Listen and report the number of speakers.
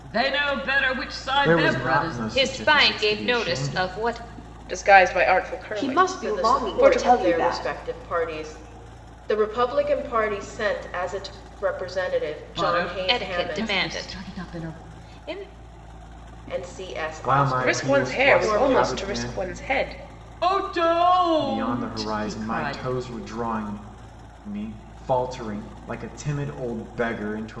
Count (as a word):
six